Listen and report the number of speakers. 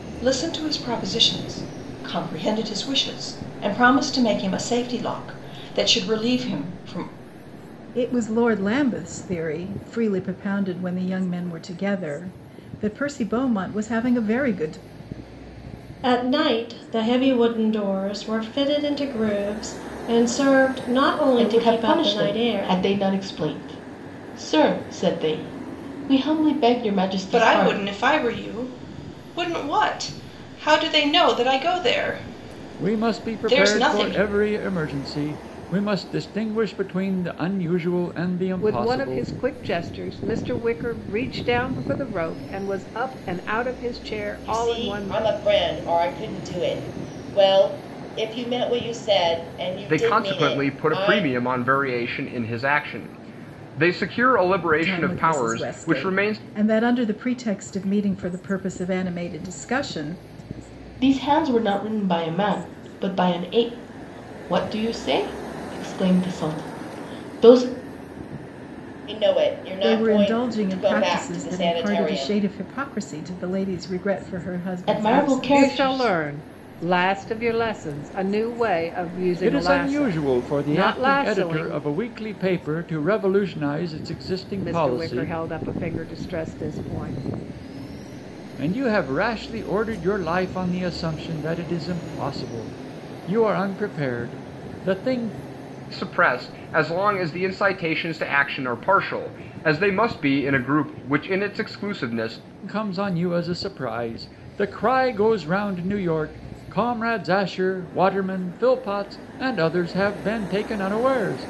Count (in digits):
9